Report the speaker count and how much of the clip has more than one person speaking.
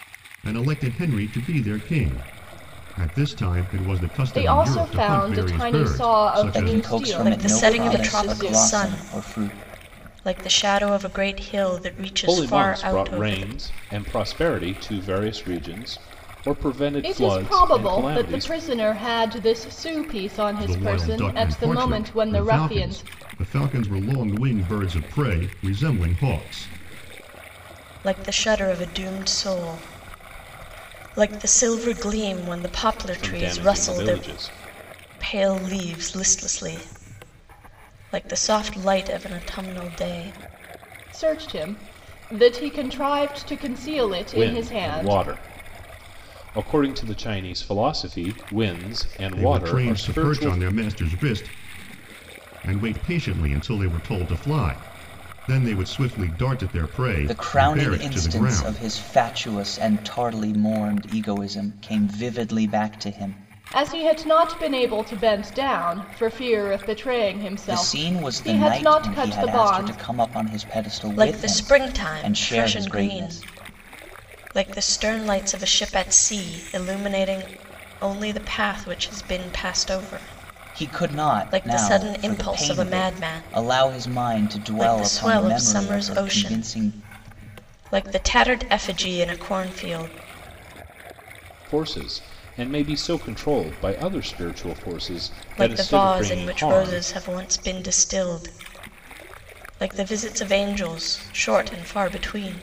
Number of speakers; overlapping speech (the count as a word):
five, about 27%